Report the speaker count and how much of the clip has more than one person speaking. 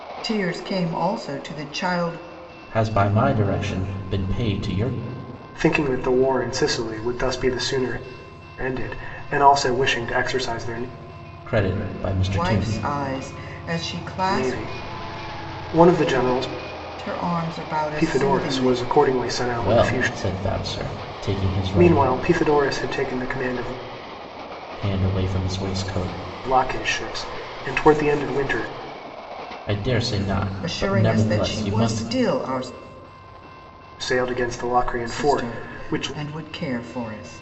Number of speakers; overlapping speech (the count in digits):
3, about 14%